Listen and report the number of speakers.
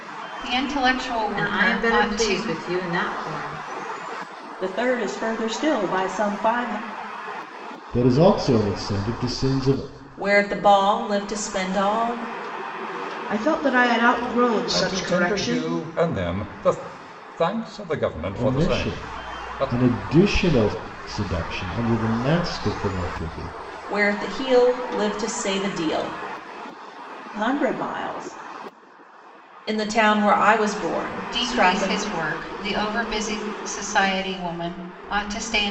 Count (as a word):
seven